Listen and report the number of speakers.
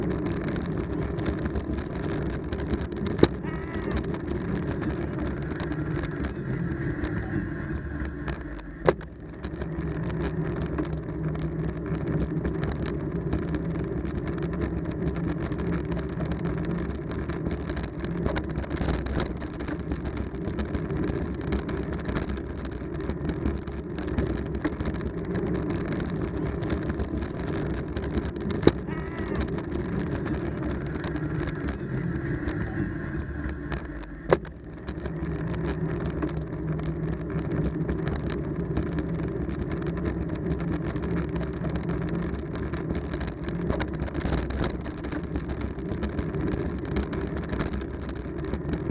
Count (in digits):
0